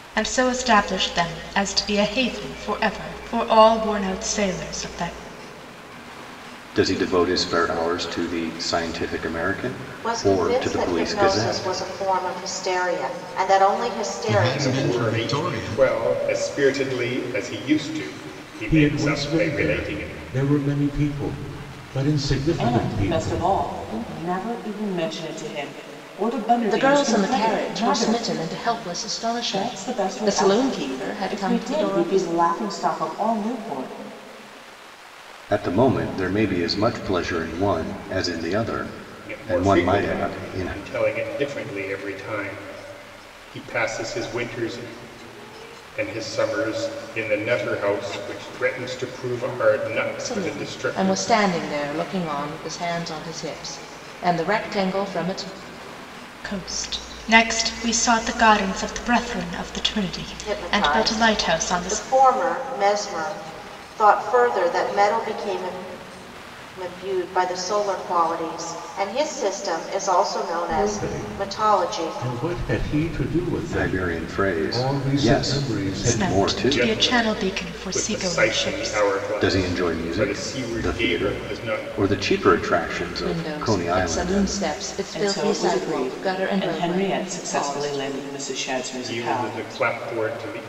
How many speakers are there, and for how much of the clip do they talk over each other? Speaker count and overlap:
8, about 32%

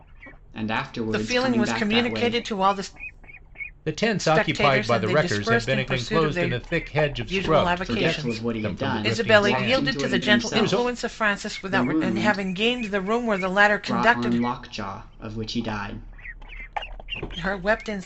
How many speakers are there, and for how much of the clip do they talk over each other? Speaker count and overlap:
3, about 52%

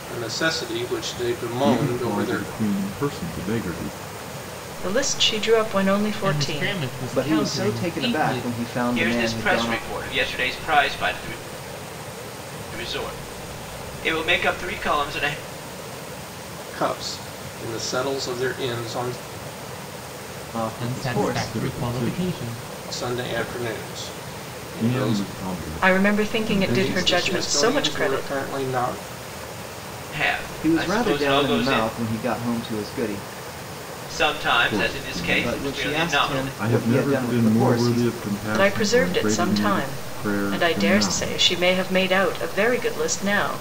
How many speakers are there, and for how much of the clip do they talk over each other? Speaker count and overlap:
6, about 40%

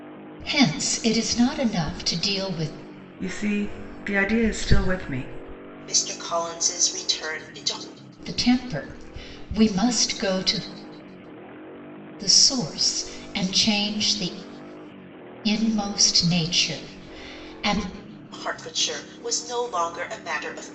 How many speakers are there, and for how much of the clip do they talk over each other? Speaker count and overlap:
3, no overlap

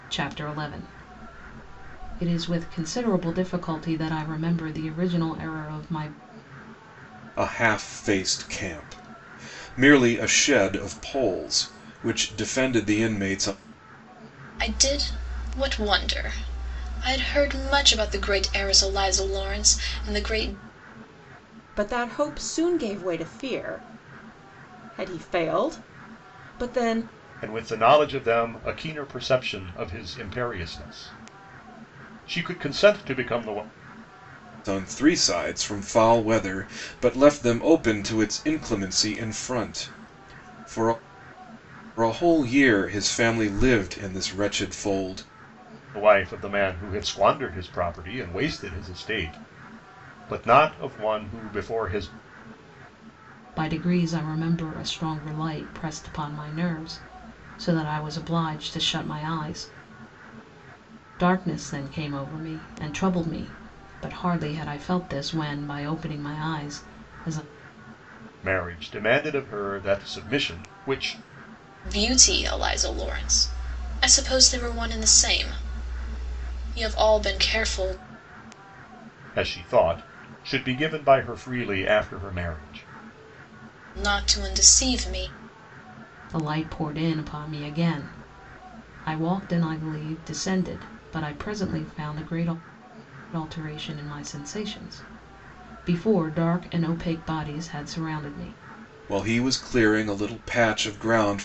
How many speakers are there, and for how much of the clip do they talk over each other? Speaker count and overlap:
5, no overlap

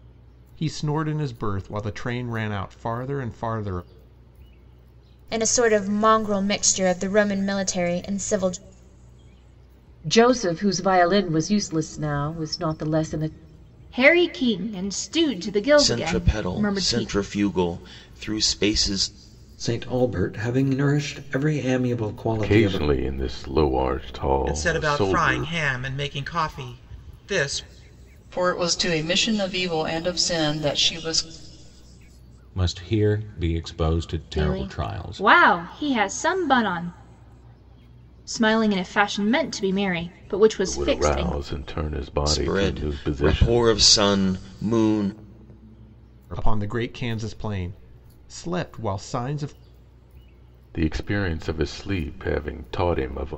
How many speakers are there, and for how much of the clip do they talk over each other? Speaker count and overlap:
10, about 11%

